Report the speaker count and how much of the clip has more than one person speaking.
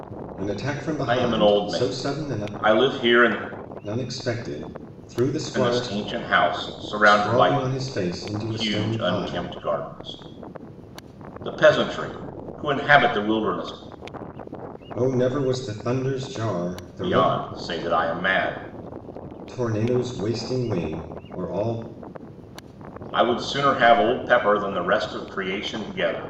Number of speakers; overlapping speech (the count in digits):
2, about 14%